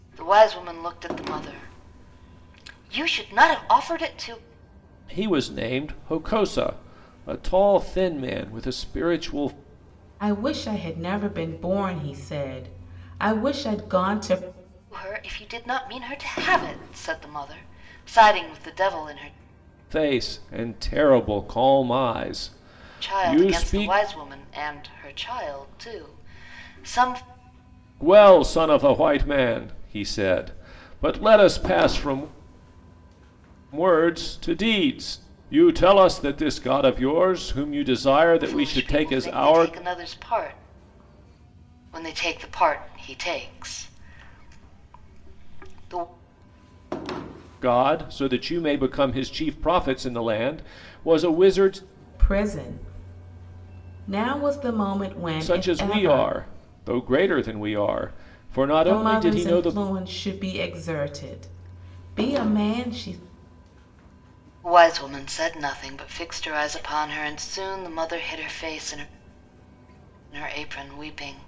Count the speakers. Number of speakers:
3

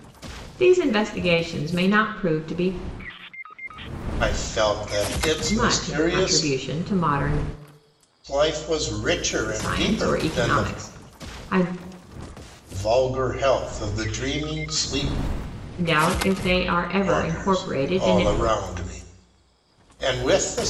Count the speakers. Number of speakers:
2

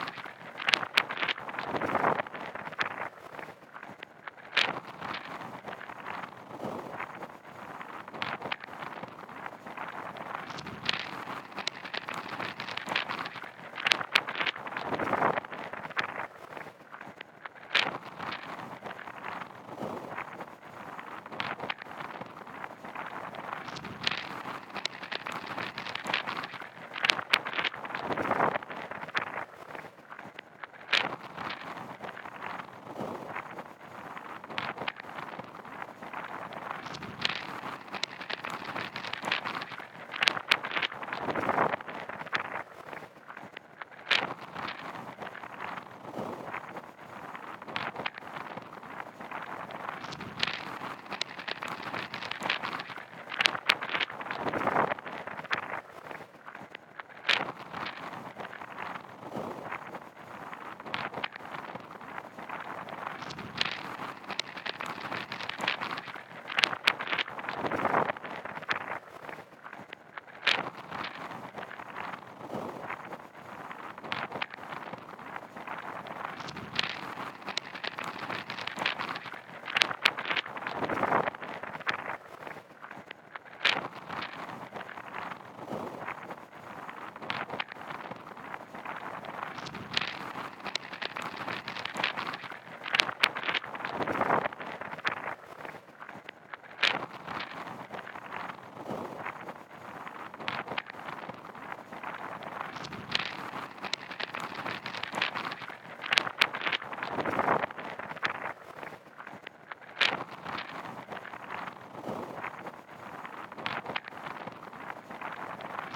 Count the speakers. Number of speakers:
0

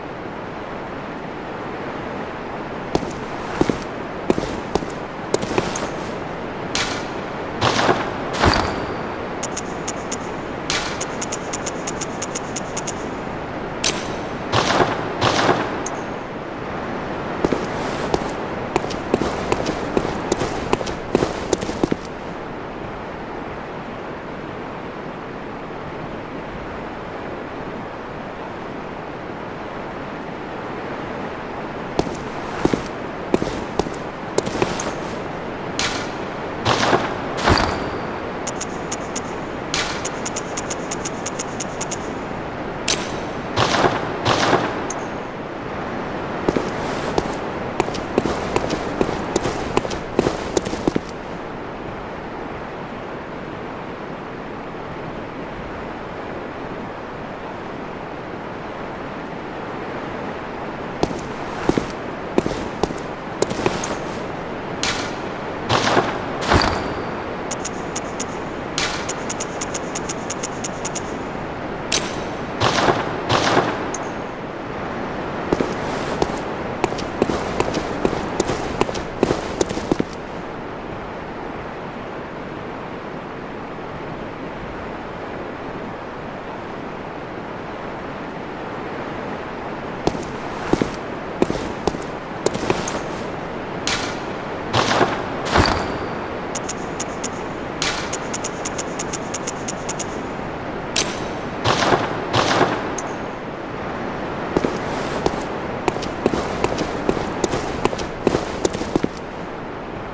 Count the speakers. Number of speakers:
0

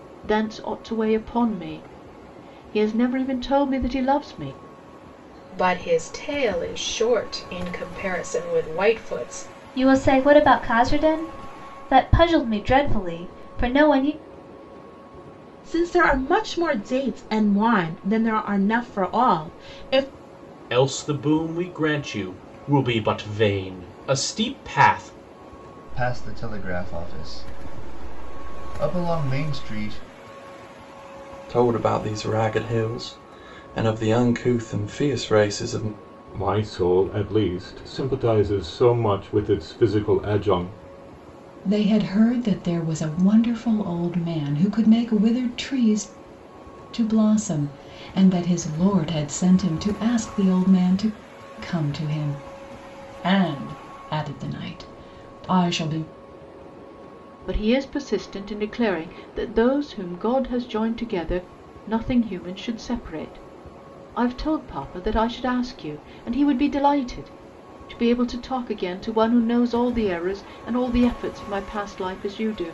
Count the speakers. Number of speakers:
9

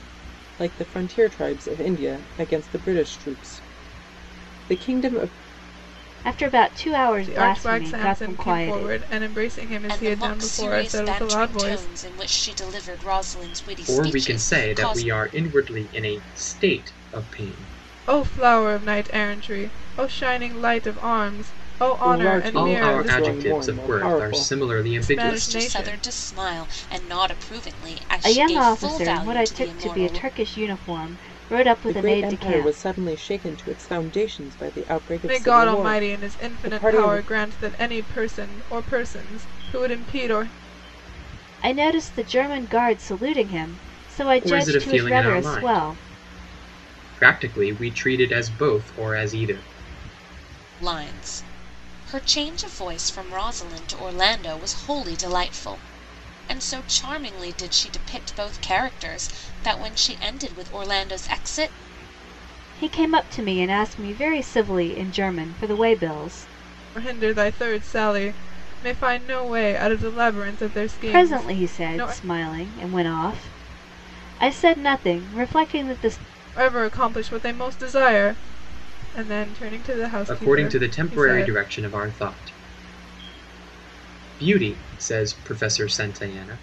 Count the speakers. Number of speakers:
5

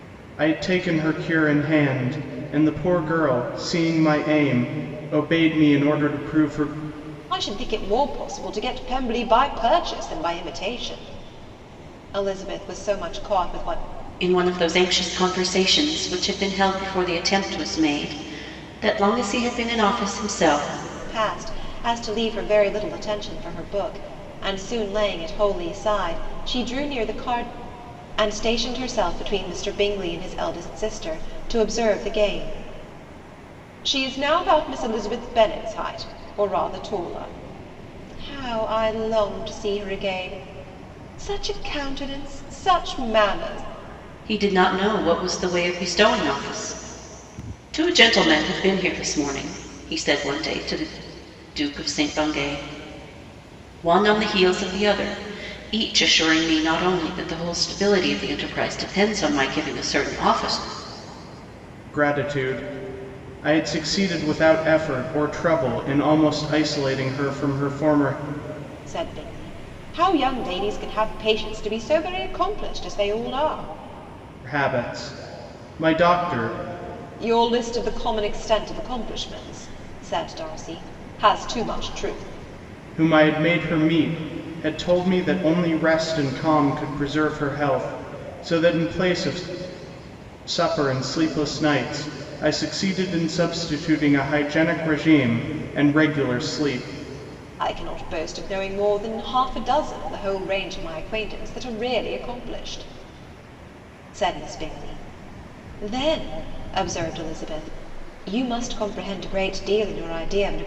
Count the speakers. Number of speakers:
3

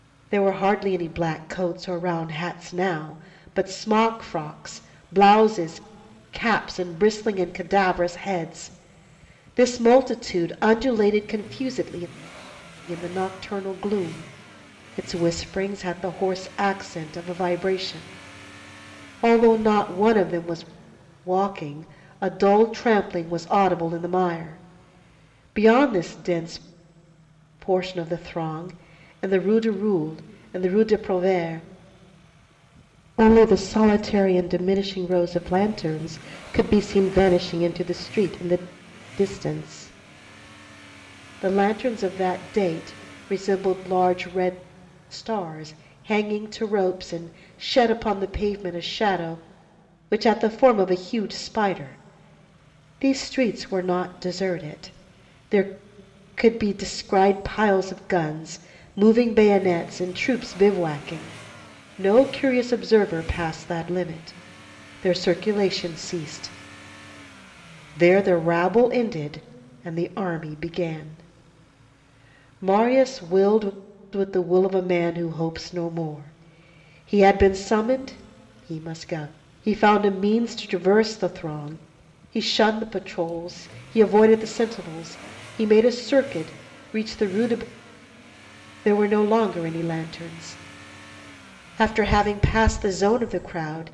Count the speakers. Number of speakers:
1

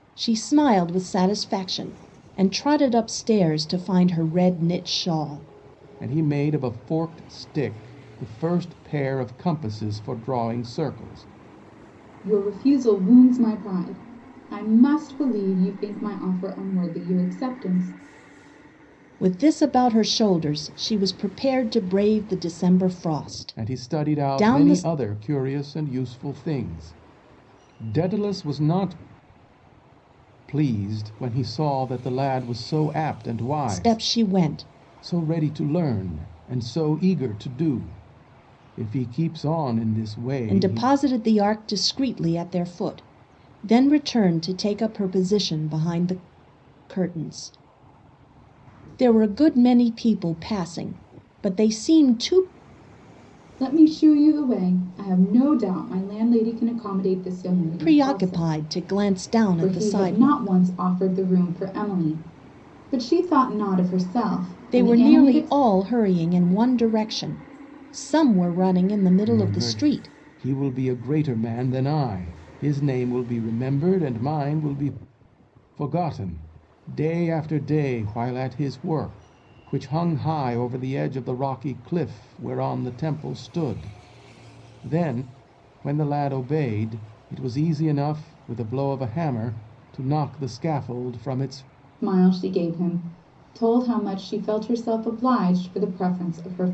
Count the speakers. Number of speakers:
3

